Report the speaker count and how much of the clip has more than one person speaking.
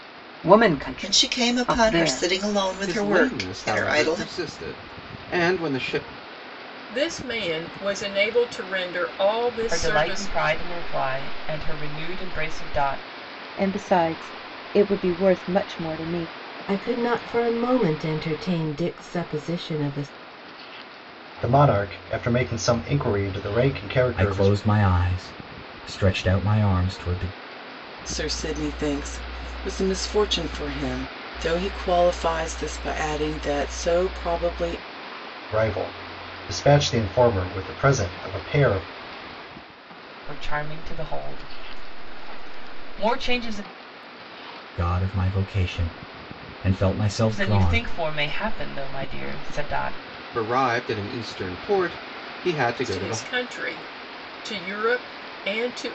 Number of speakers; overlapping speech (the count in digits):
10, about 9%